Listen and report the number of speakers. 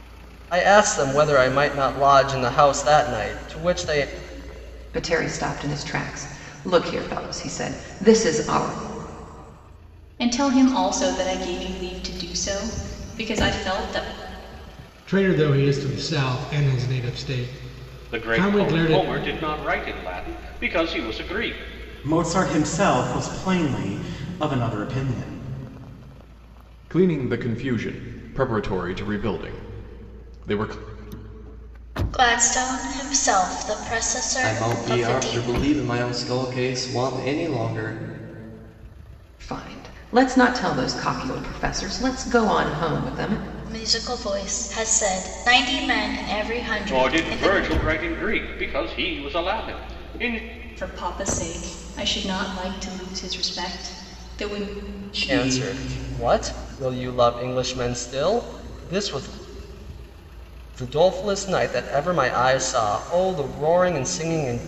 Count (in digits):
9